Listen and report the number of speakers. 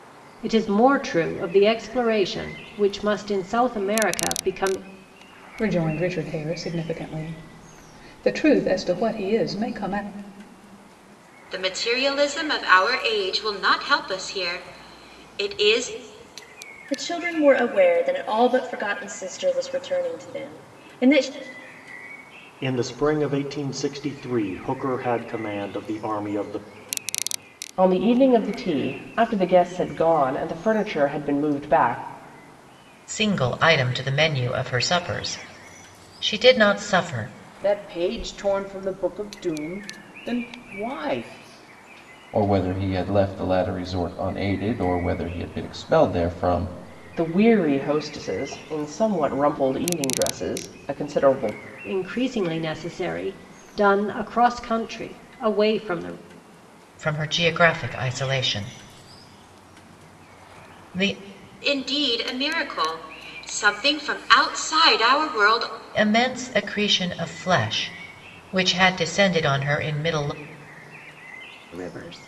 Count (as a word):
nine